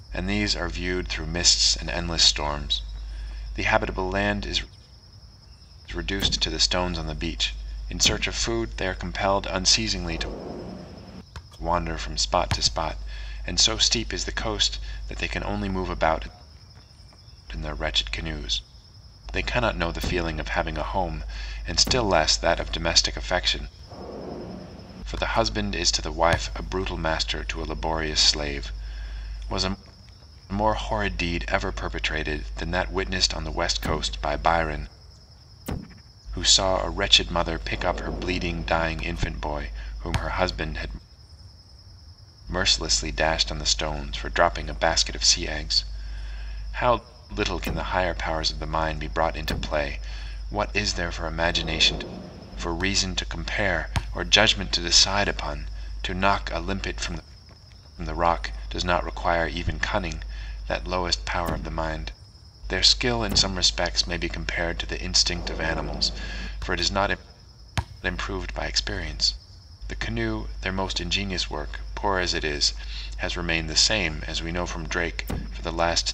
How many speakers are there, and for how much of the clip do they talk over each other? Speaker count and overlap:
one, no overlap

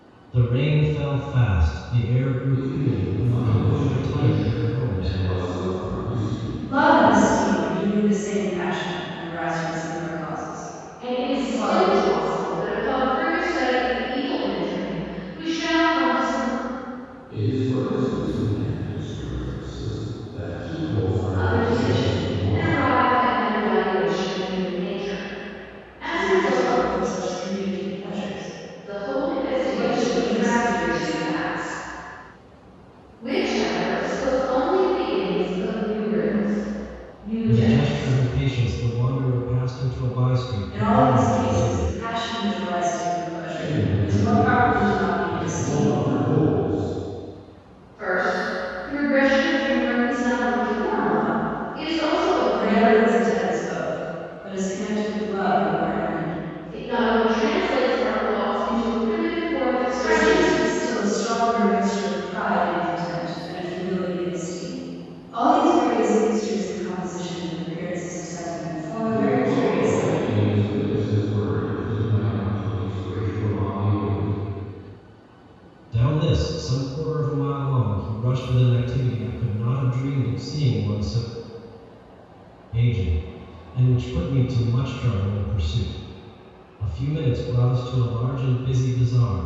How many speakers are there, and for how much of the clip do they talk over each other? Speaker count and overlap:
four, about 21%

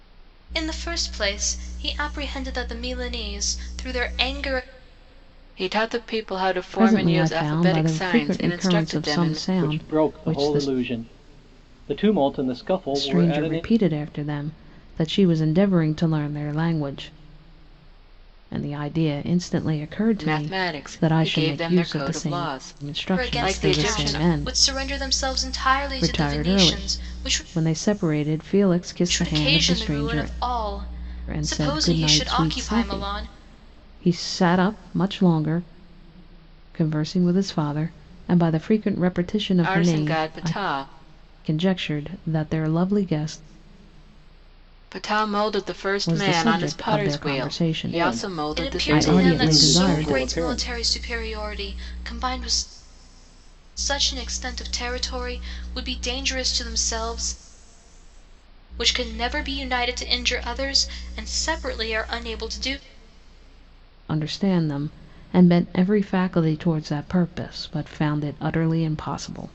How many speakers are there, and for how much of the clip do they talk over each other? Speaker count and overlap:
four, about 28%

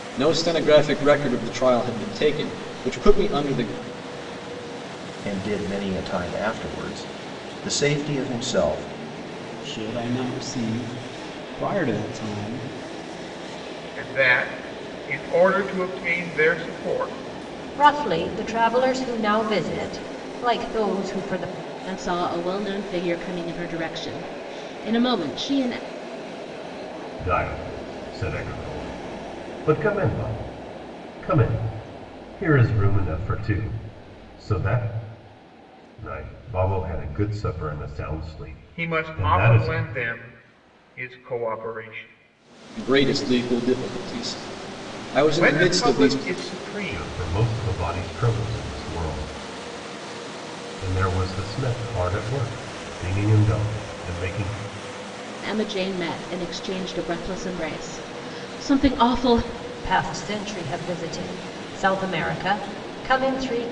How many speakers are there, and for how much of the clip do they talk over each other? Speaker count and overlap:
seven, about 4%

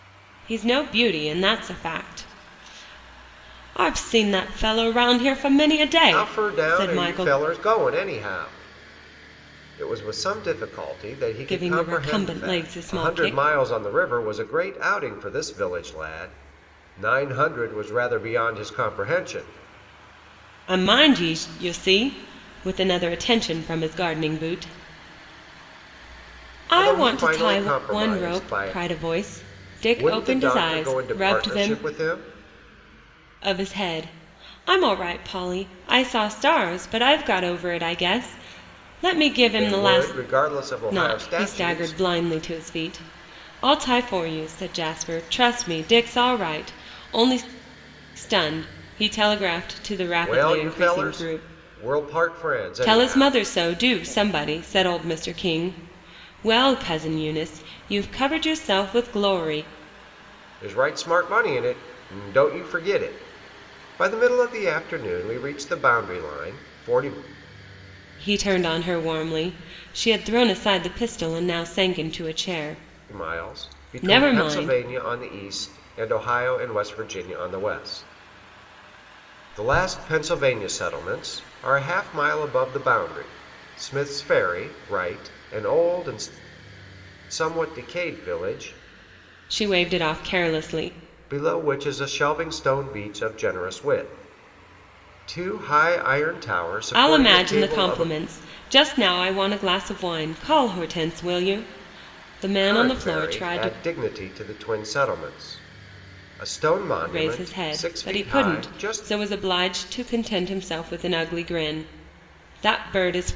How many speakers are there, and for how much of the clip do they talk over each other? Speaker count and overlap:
two, about 15%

